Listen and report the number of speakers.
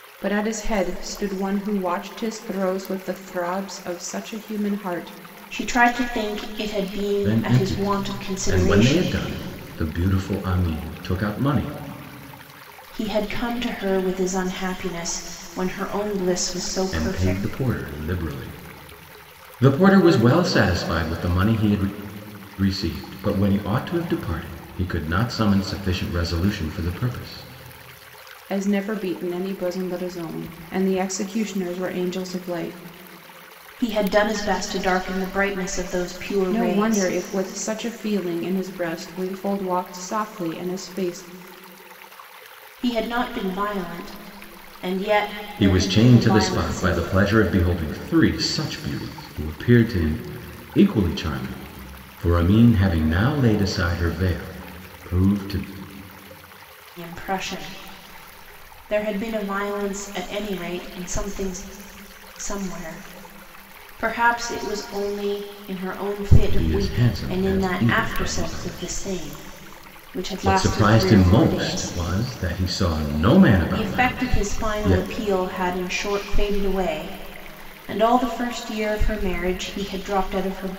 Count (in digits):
3